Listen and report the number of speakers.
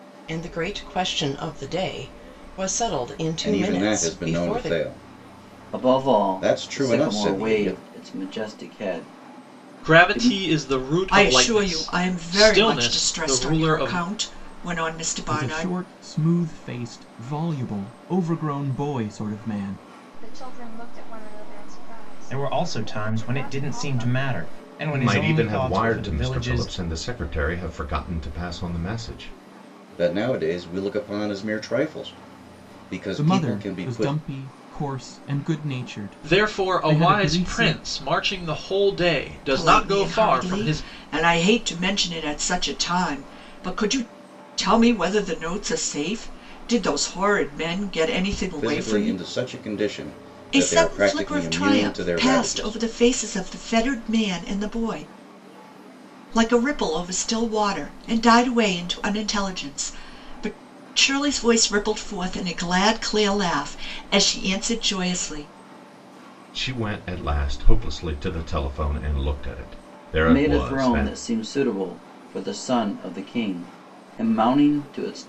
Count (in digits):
9